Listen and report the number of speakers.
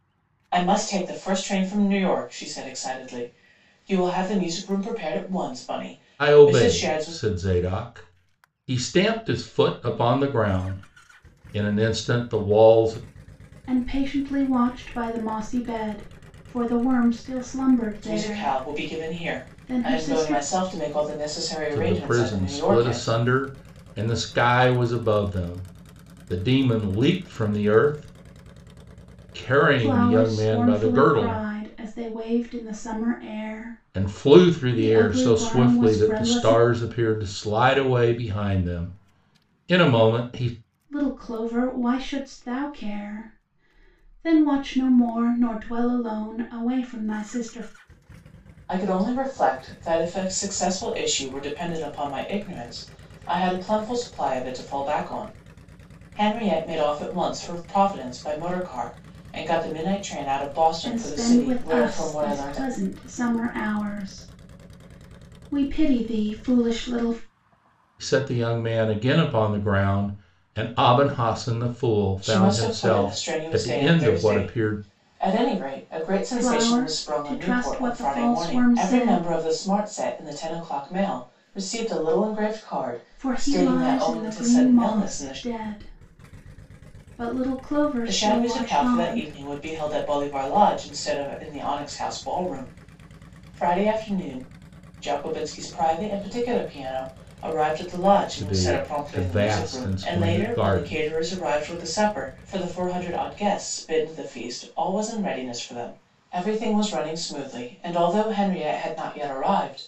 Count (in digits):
3